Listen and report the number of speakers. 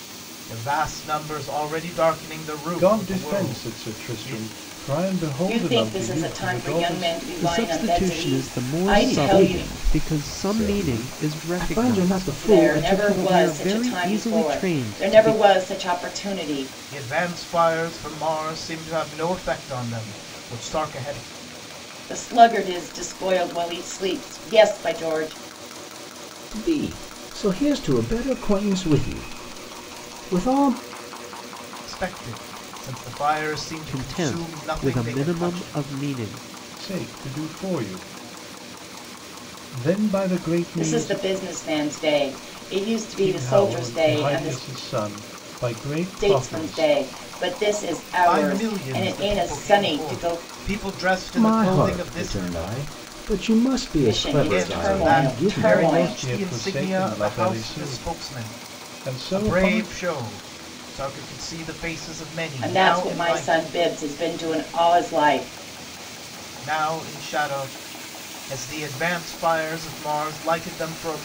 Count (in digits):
5